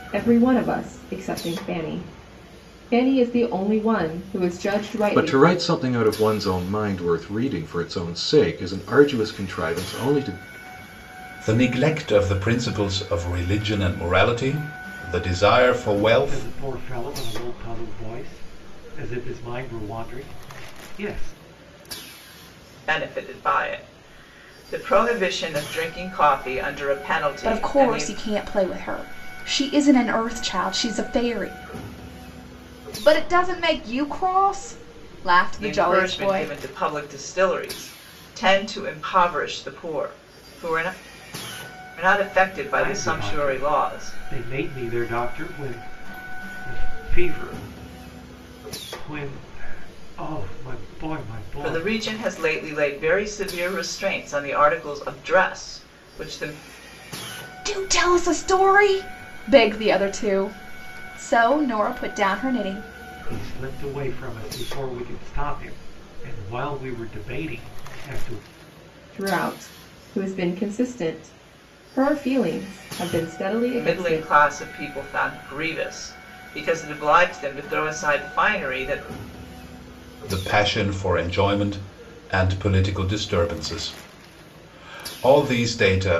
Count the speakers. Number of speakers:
six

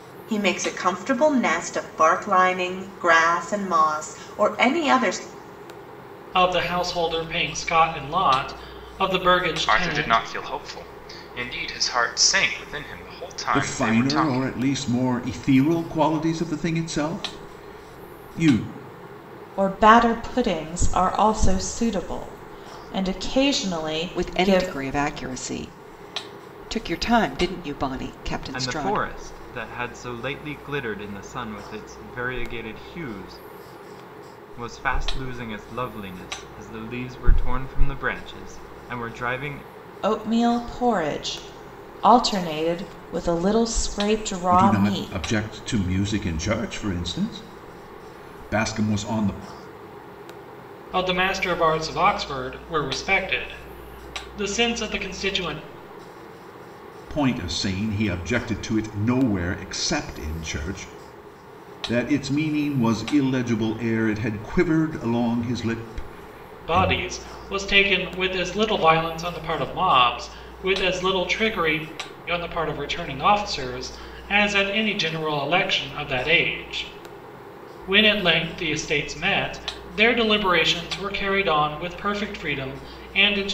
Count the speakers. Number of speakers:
seven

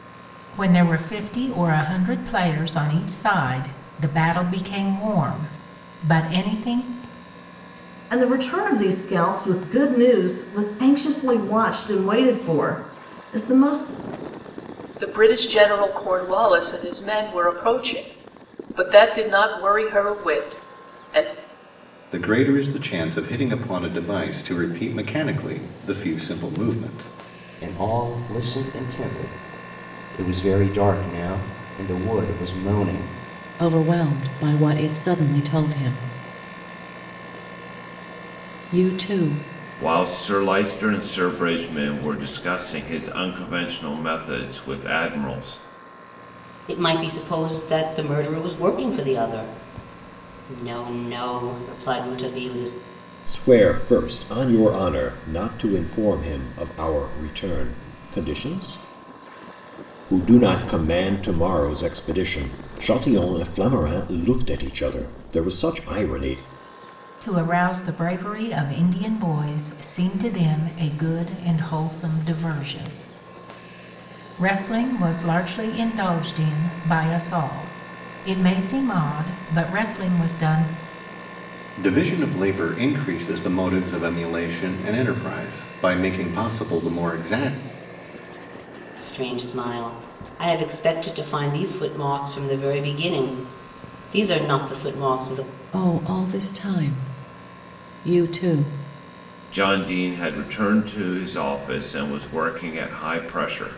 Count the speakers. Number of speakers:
nine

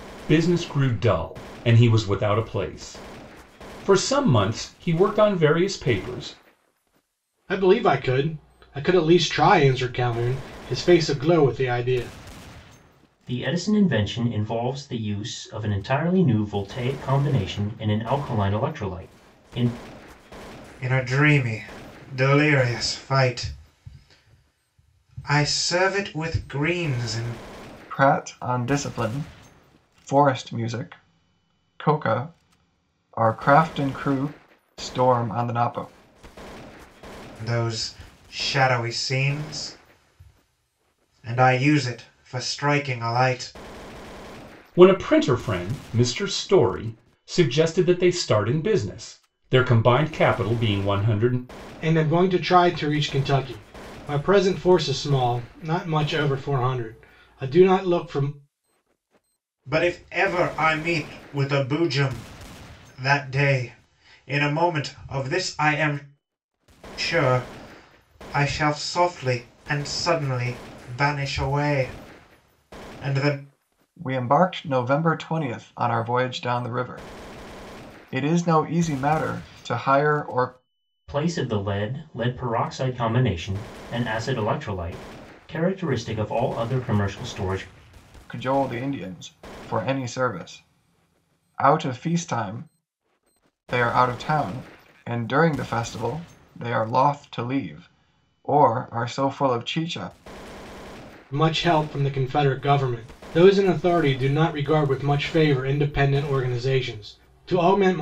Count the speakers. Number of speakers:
five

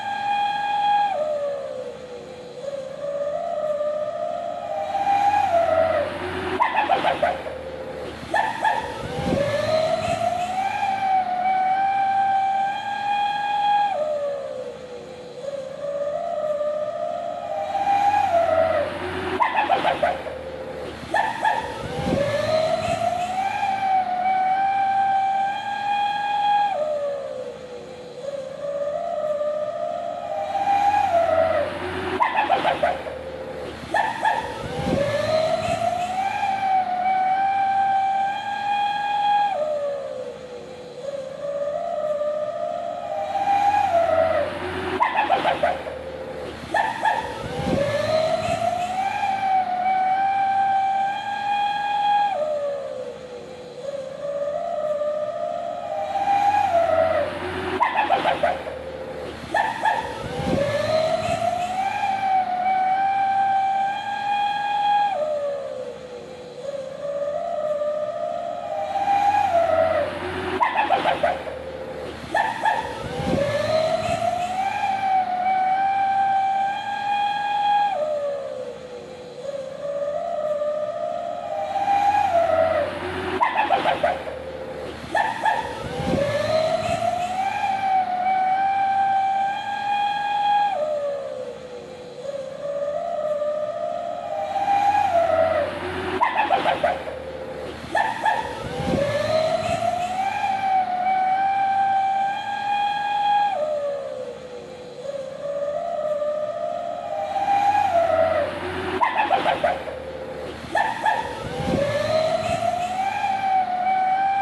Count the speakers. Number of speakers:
zero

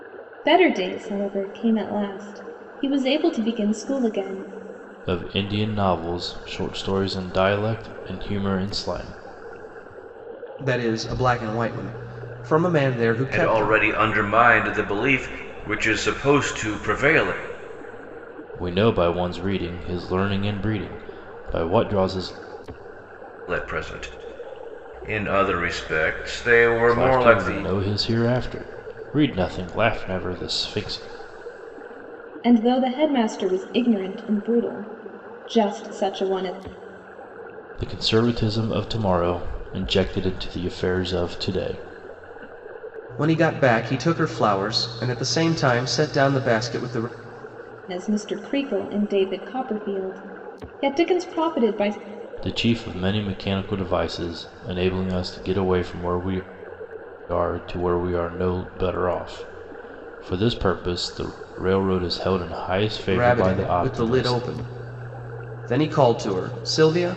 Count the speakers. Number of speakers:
four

